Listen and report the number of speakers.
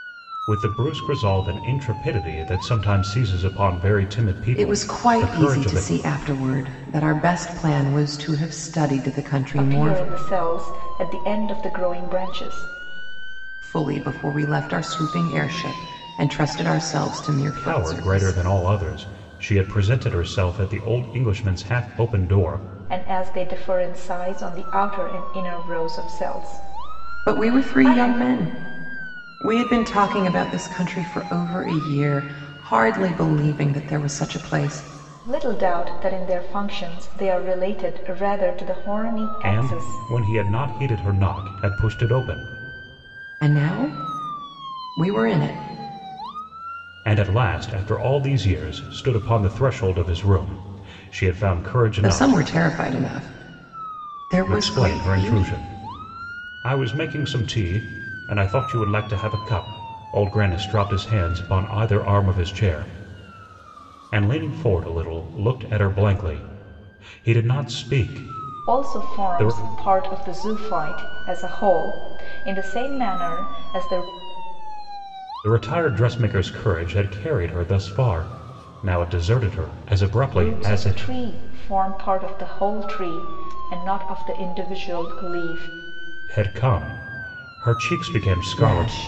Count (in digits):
3